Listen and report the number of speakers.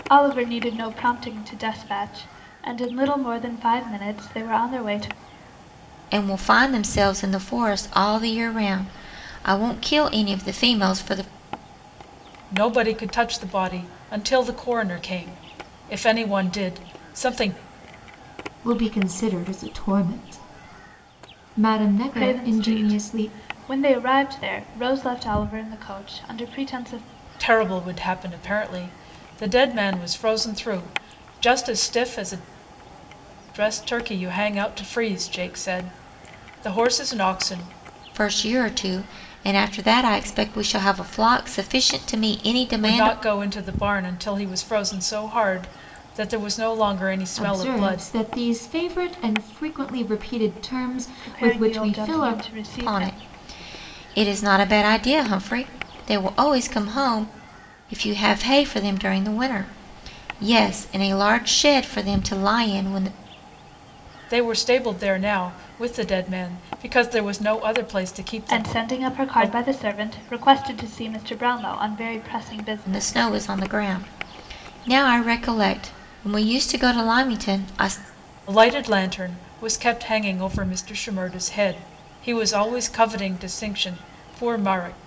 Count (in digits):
4